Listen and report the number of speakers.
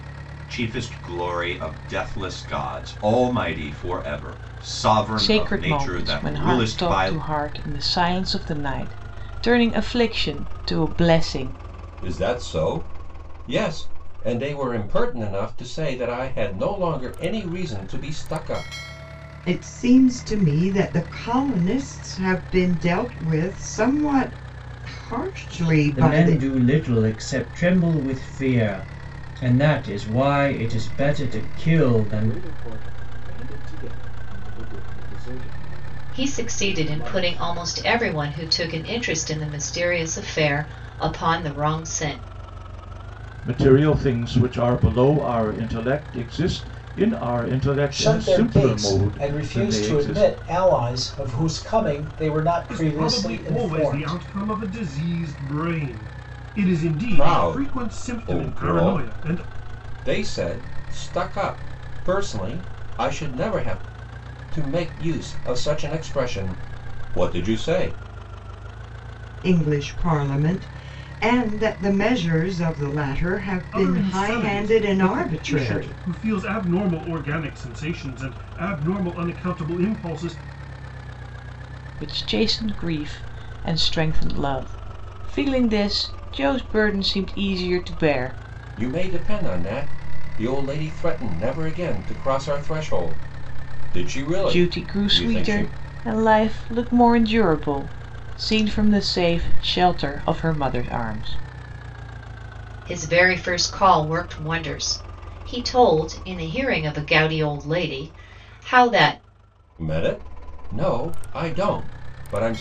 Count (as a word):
ten